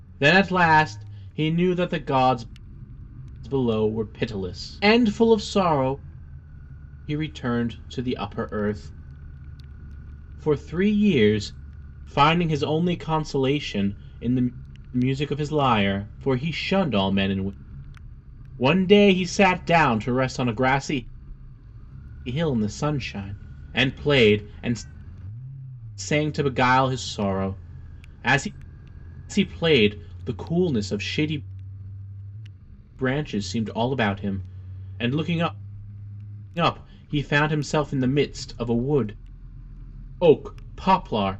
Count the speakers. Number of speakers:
1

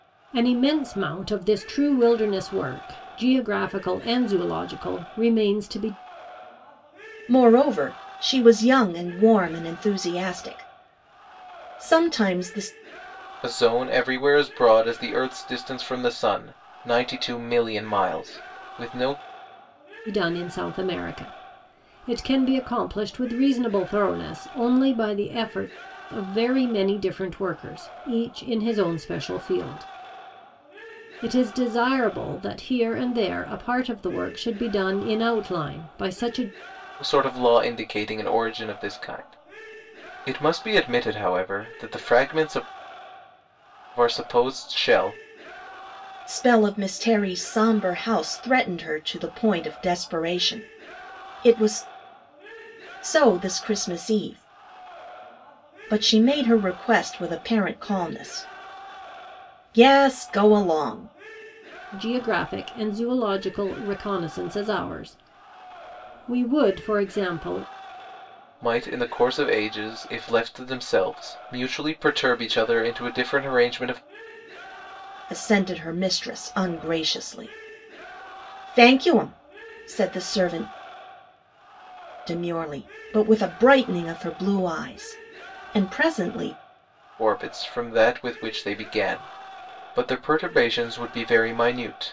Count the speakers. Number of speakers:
3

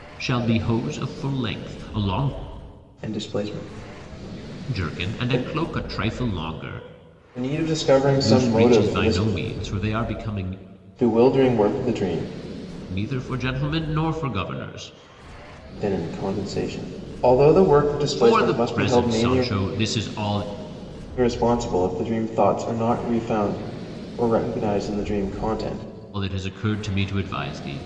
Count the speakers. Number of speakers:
2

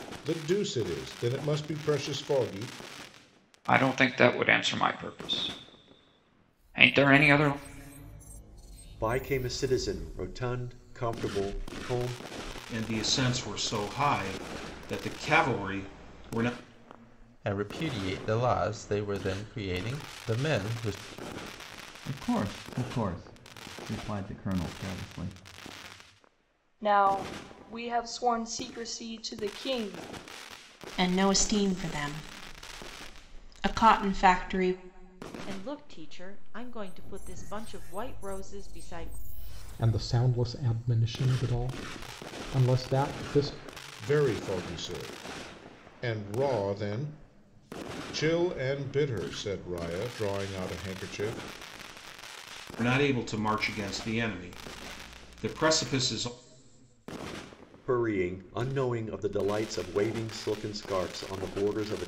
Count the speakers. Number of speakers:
10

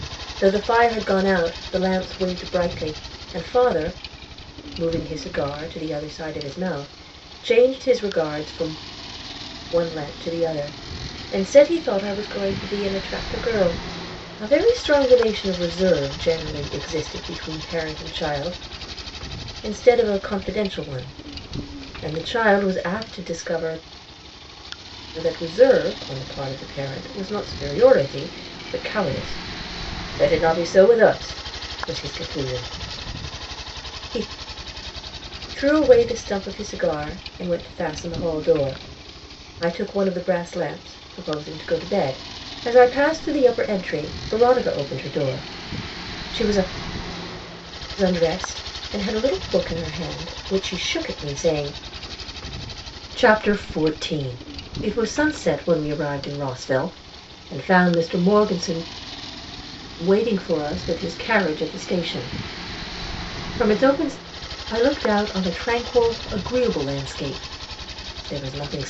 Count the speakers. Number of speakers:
1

